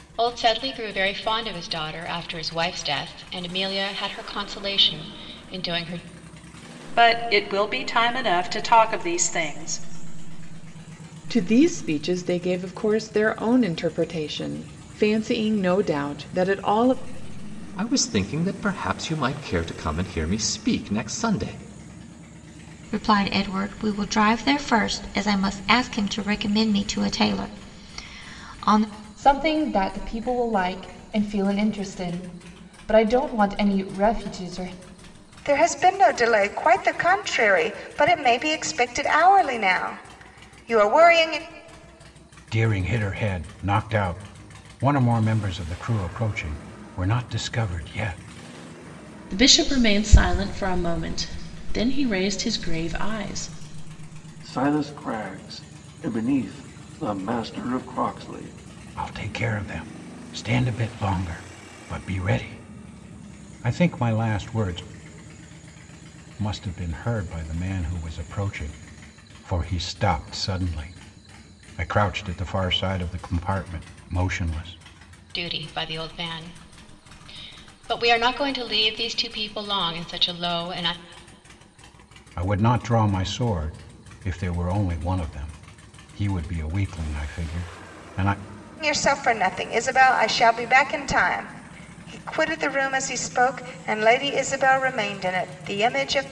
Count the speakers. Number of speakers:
10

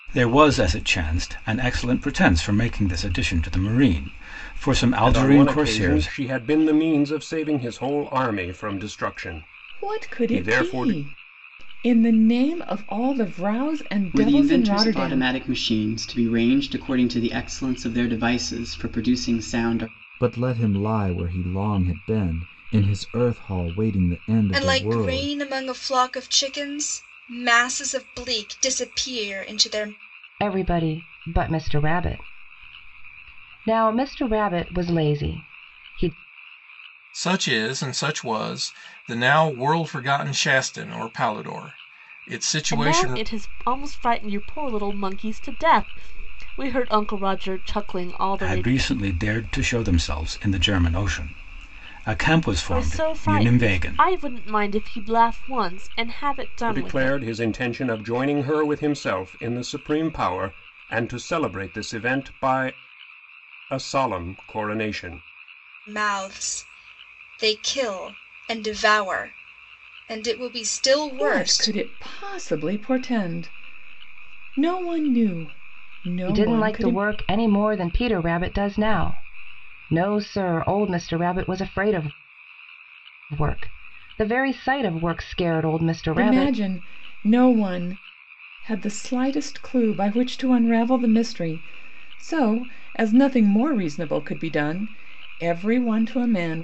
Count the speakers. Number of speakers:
9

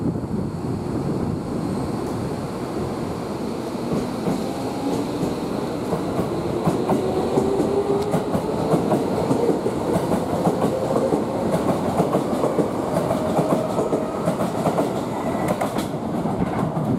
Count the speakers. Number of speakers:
0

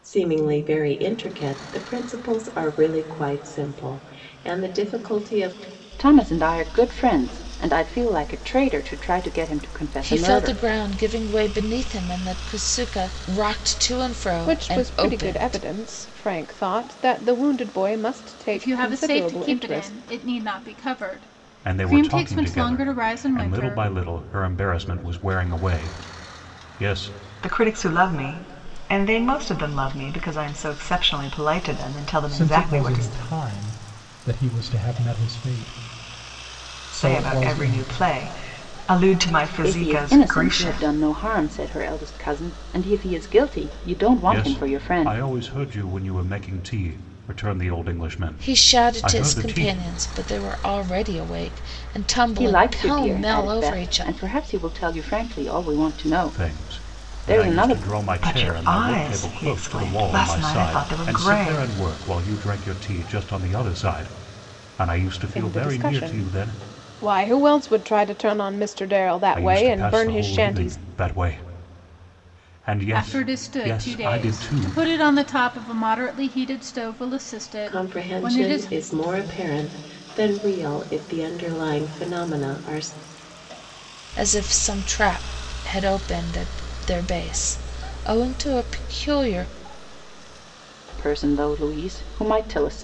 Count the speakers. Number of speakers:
8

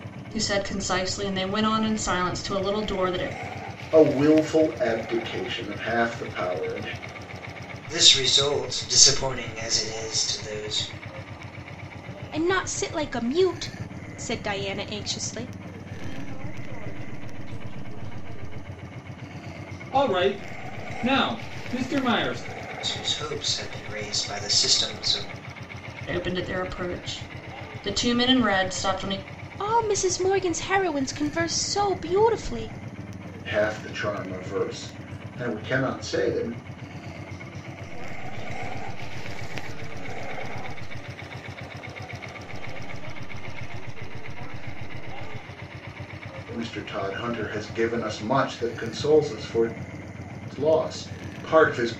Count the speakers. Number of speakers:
6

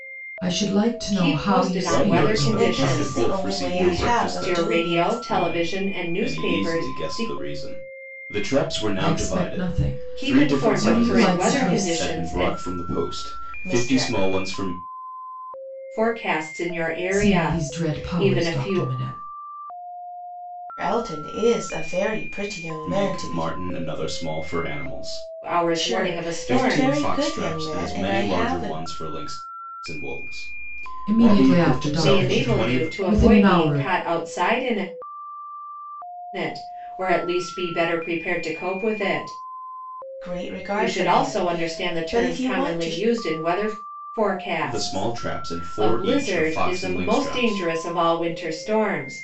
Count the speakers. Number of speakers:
4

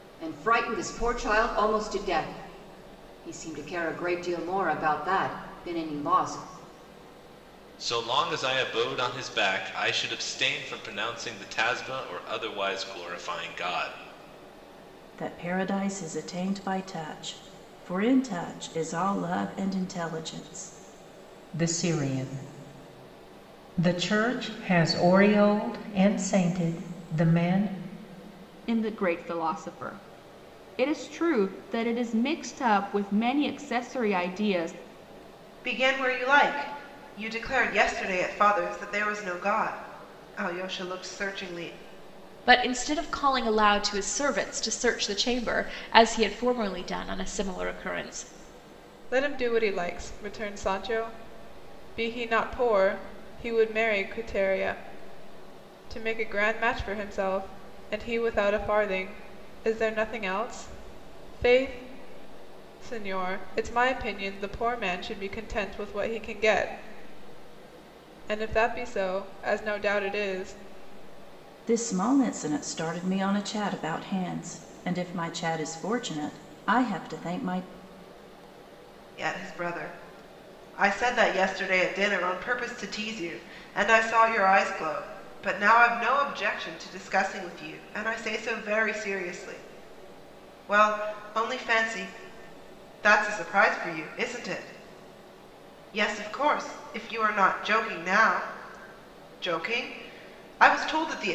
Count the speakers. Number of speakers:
8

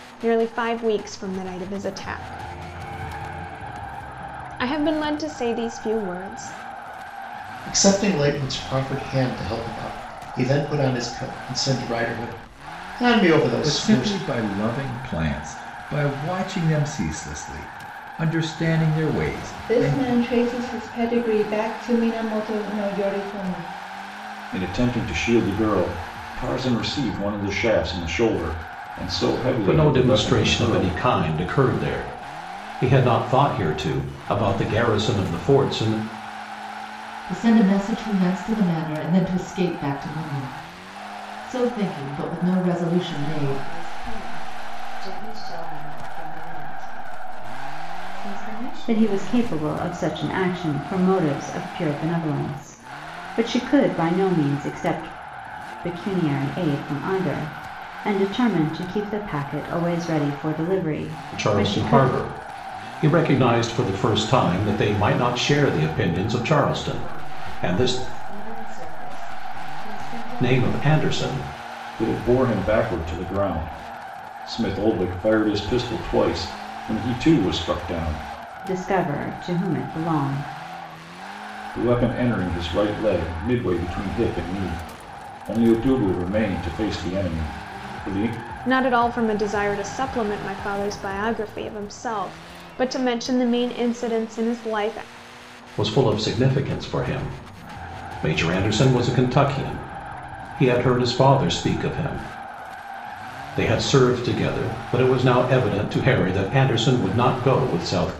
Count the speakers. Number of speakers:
9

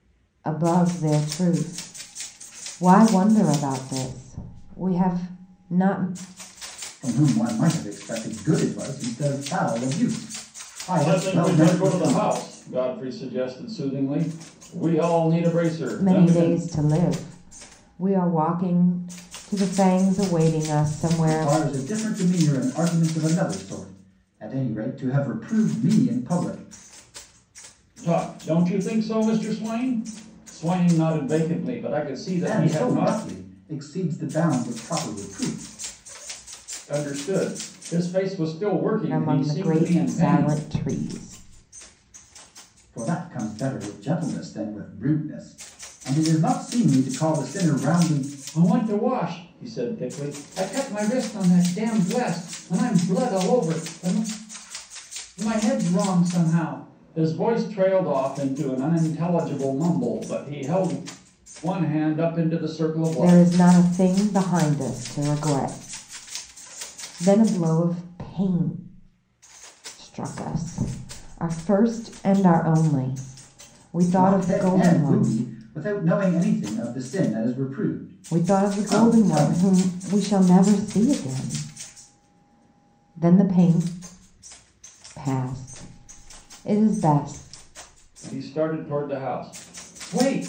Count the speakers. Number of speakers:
3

